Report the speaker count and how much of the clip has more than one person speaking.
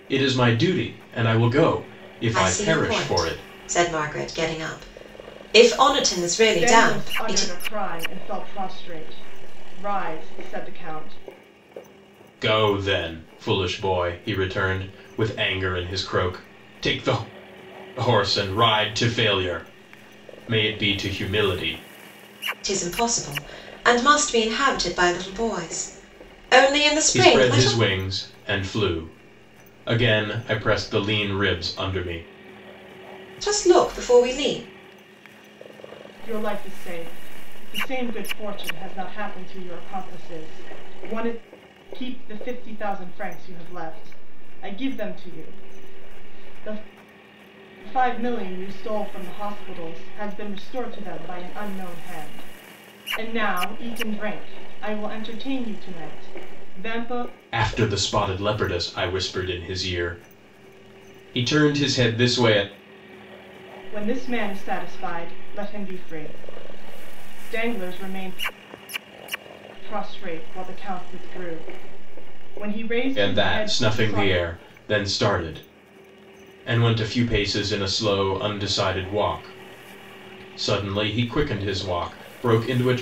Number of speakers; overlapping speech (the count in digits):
3, about 5%